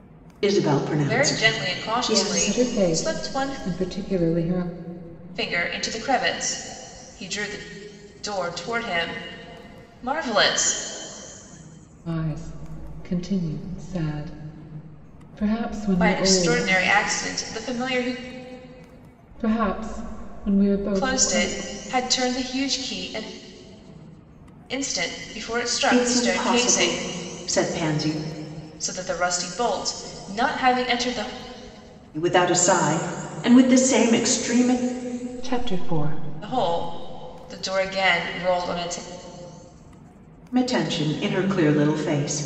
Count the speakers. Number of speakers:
3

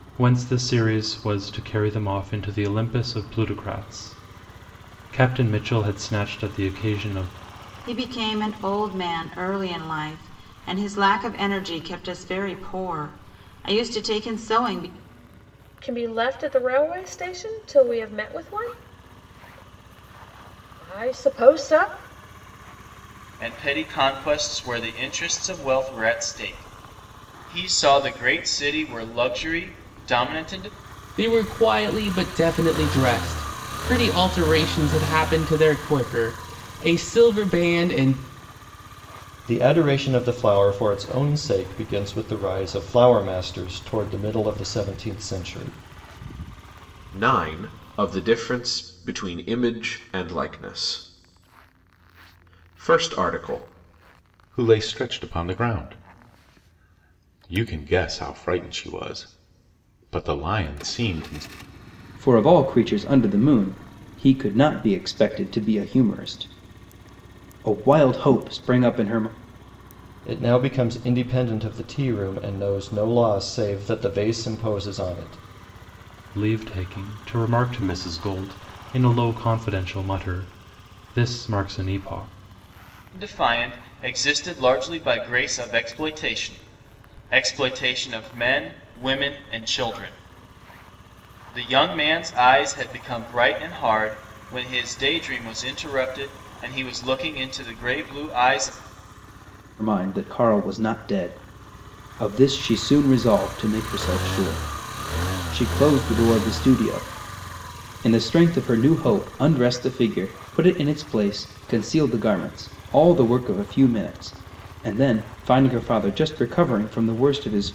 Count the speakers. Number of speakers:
9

